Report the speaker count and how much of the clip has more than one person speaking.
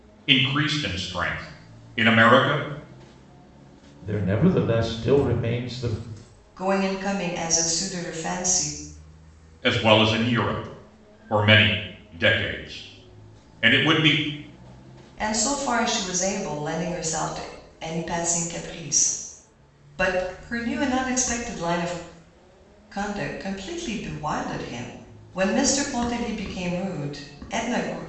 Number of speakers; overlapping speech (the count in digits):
3, no overlap